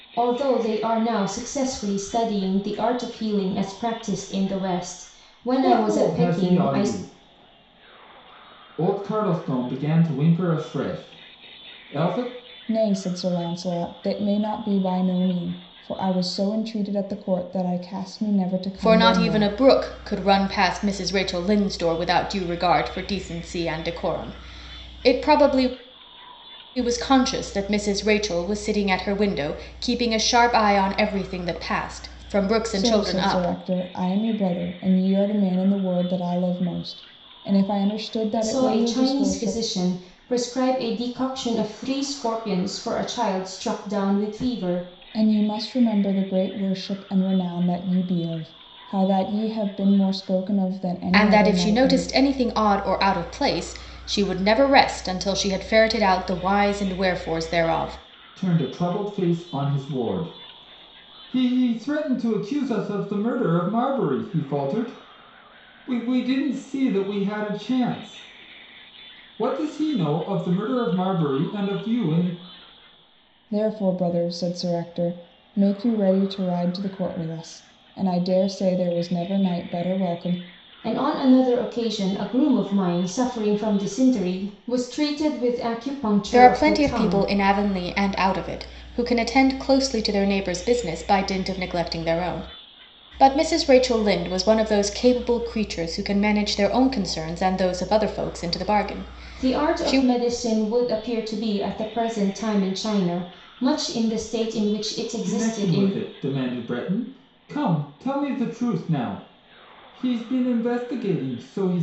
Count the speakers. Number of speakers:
four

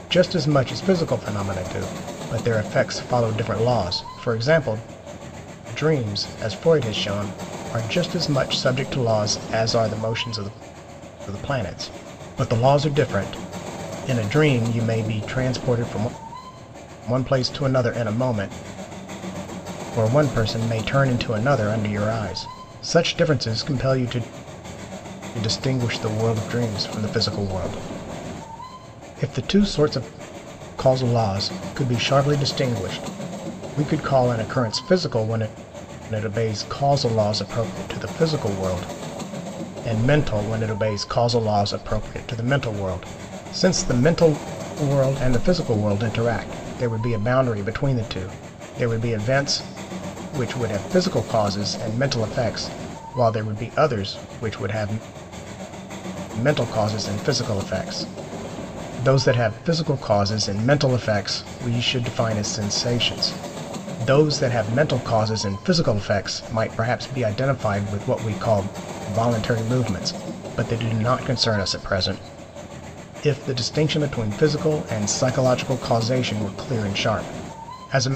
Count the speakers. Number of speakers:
one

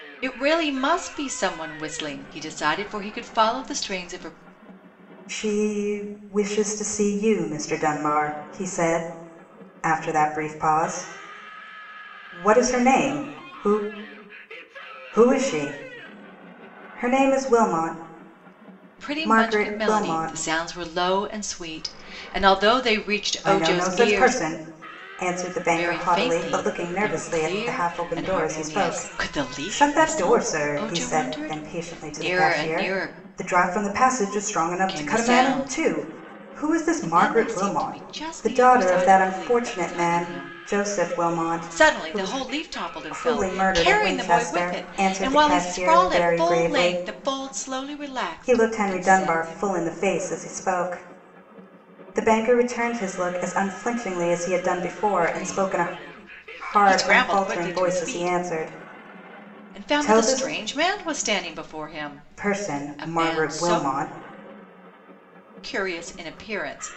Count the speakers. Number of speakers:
two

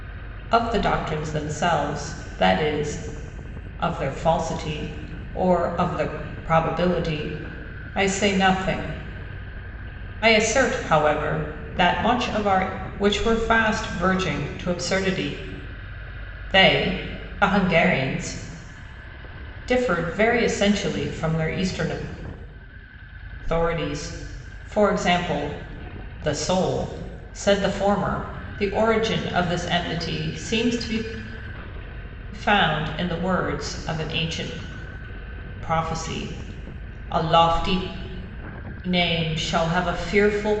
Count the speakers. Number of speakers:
one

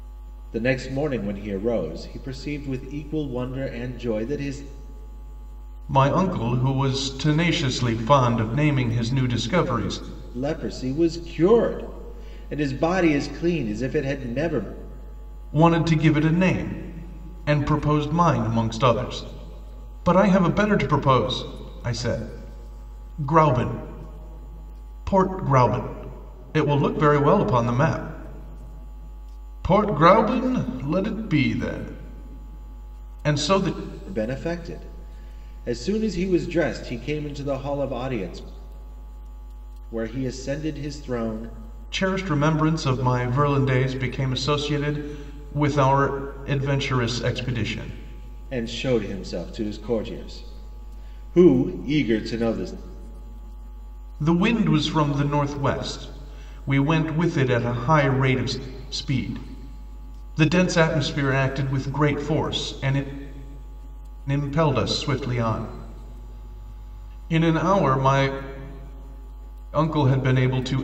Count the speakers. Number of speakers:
two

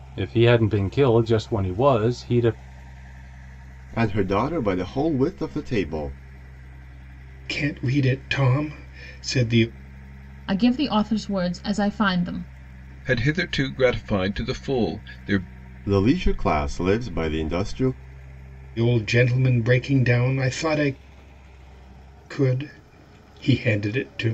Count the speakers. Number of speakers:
five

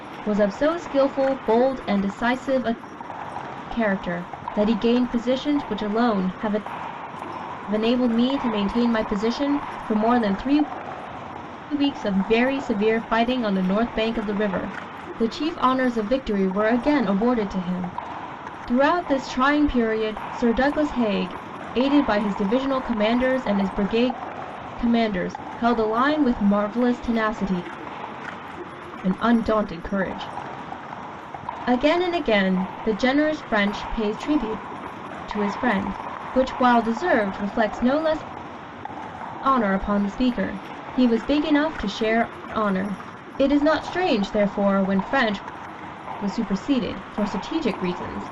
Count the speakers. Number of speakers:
one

